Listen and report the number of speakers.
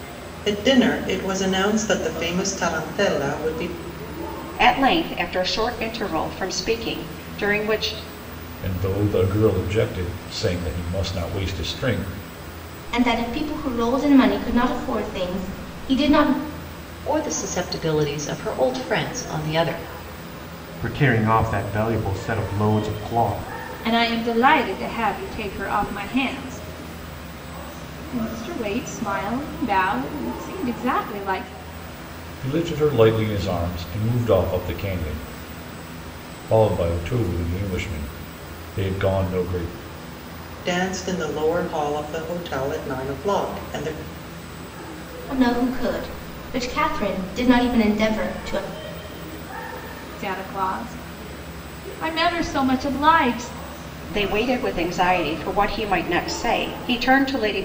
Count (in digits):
7